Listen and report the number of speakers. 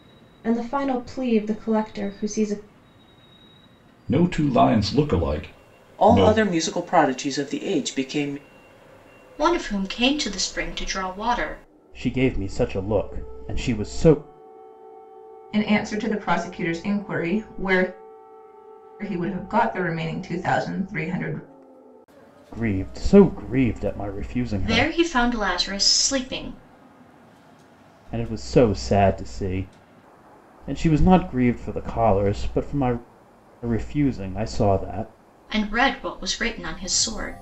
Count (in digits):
6